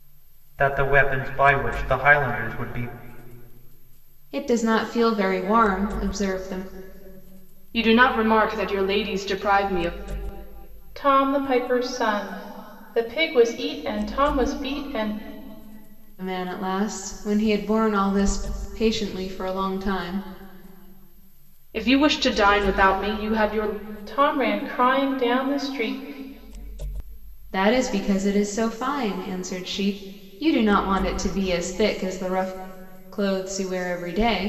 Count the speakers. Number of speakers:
four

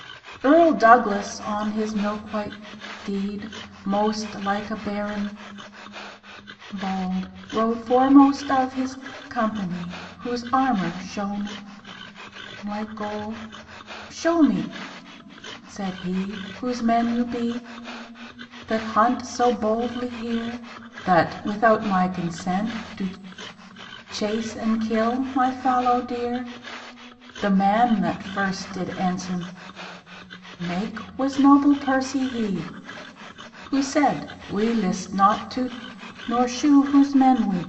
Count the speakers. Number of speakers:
one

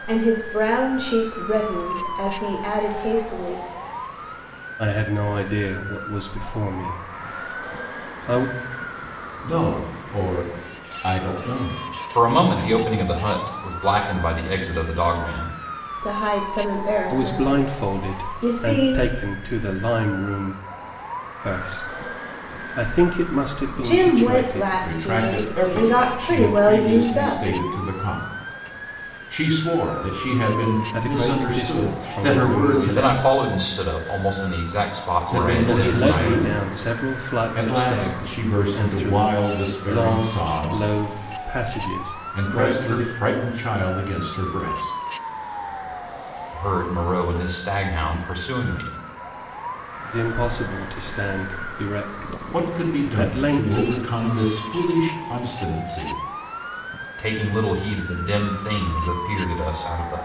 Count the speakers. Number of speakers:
four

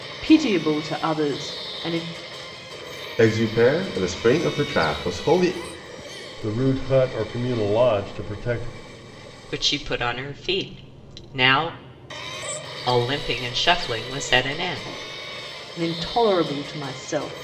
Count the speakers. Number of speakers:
four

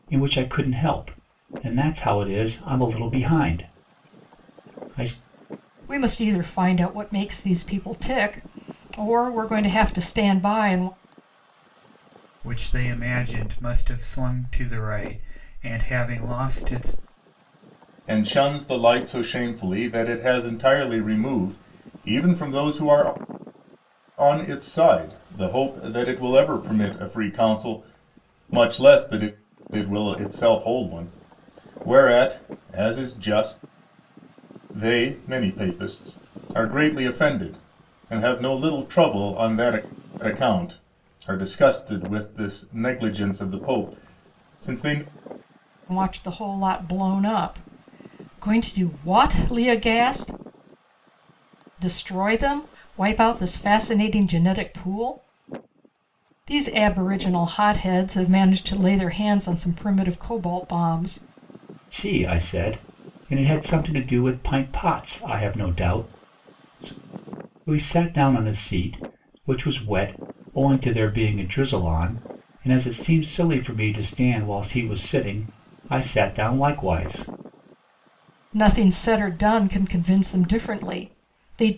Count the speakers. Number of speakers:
four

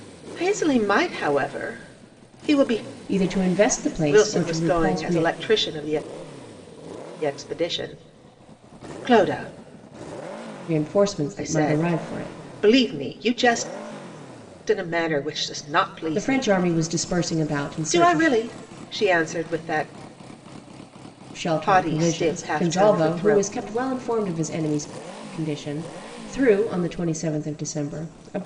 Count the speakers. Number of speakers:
two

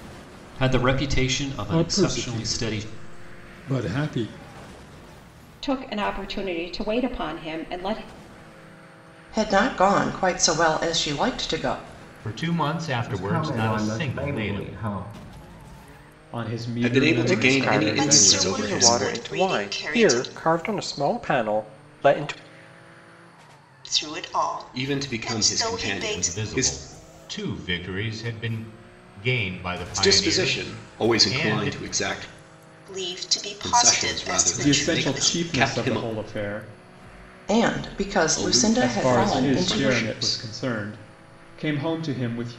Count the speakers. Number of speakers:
ten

